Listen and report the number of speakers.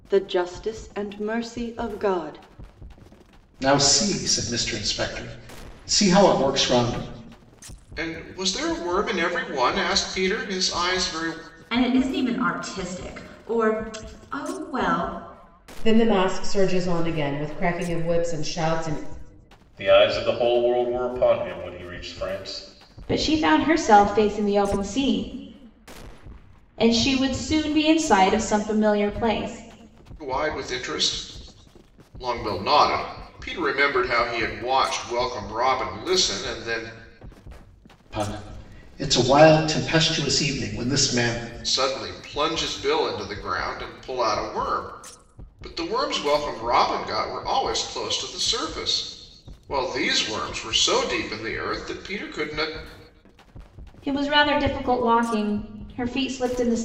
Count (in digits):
7